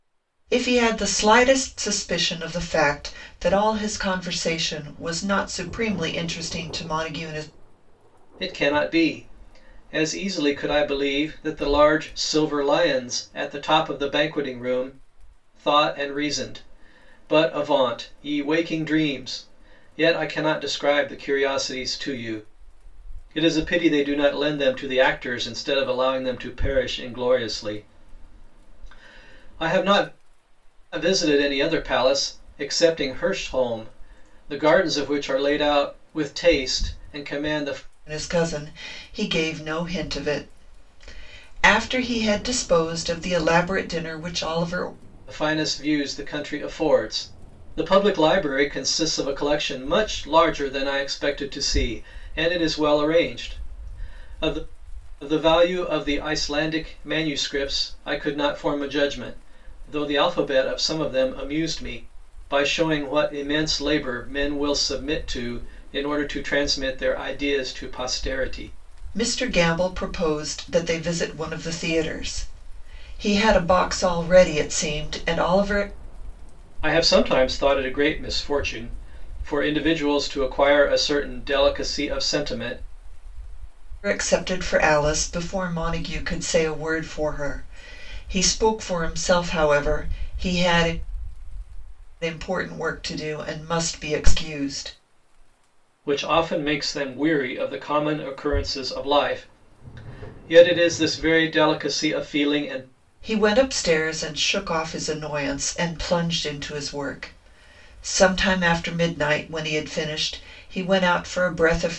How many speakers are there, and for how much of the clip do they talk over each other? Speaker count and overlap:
2, no overlap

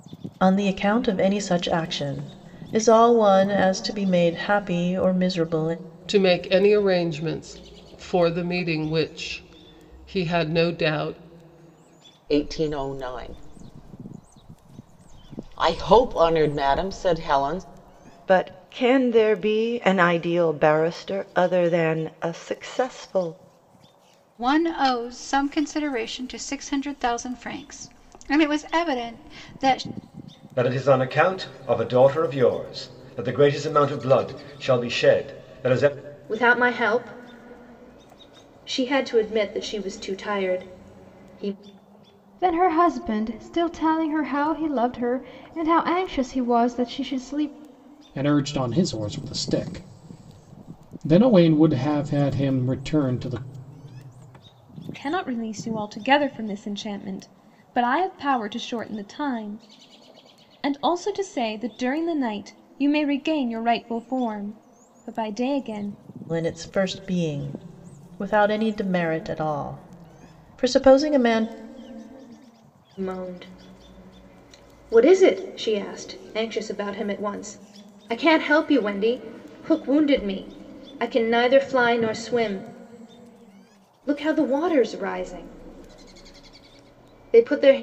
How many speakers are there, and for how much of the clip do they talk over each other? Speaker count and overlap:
10, no overlap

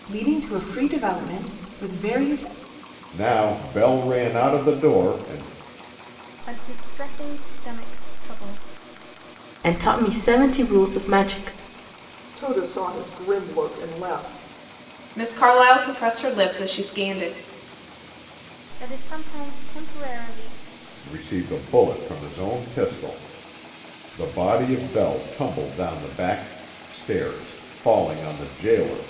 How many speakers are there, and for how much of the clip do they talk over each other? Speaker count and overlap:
6, no overlap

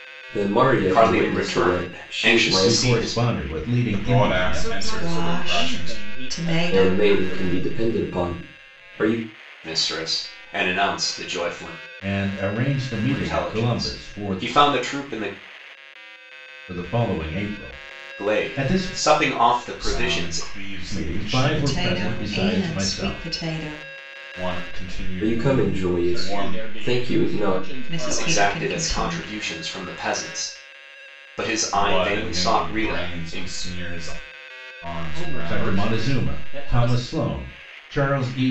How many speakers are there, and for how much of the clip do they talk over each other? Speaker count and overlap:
6, about 50%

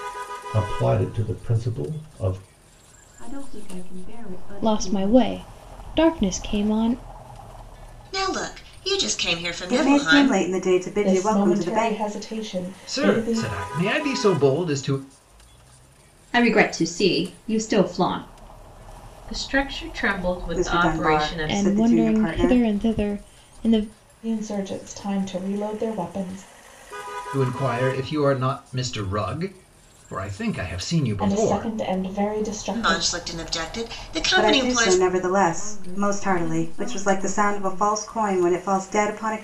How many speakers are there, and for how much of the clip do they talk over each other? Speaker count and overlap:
9, about 23%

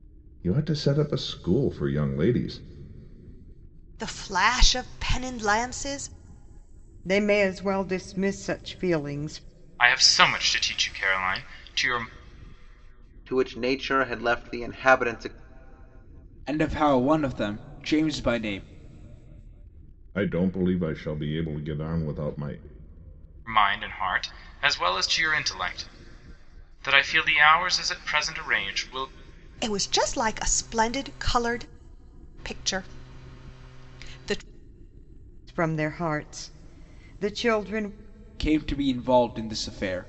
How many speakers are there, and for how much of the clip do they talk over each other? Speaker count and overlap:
6, no overlap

